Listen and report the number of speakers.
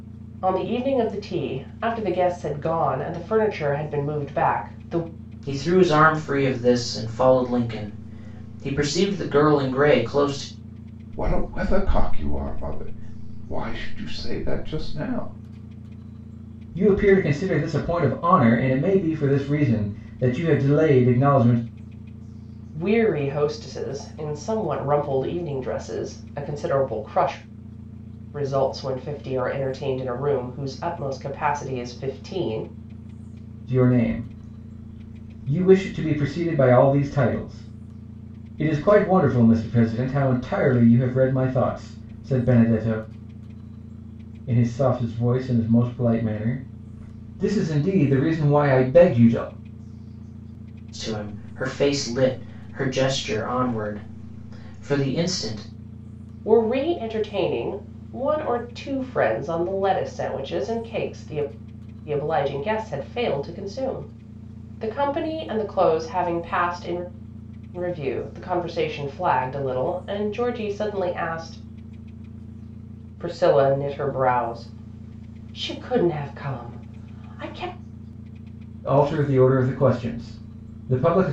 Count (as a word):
four